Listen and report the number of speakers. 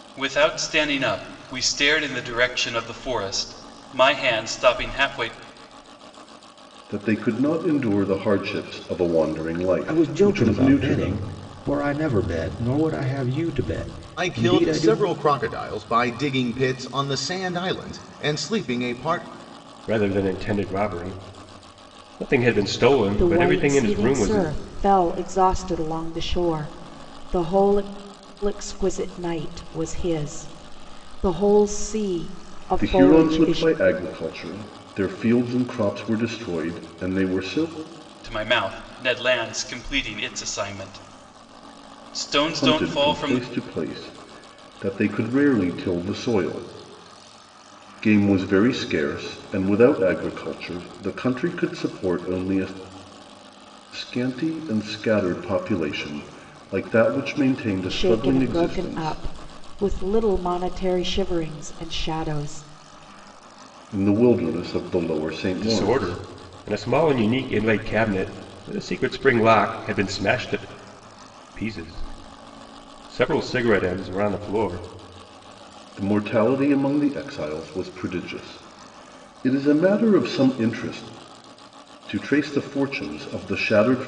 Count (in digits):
6